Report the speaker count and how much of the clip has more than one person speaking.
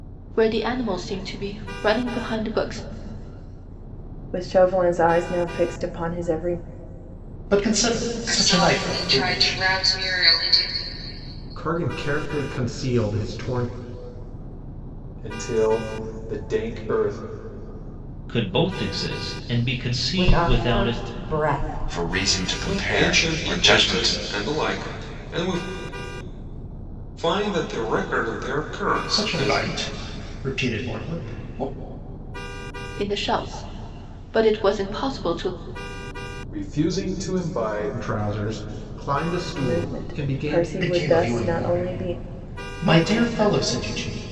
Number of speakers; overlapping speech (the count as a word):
ten, about 18%